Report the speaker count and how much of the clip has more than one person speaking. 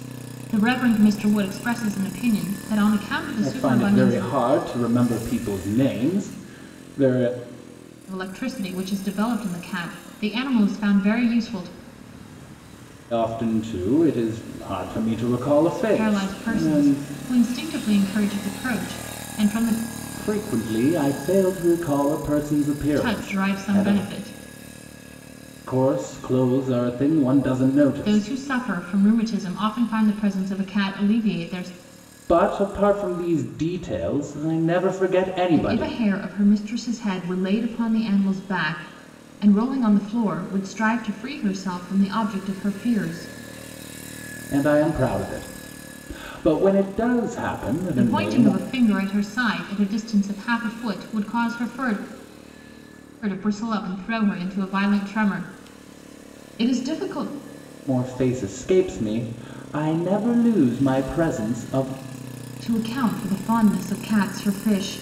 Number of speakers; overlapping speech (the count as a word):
two, about 7%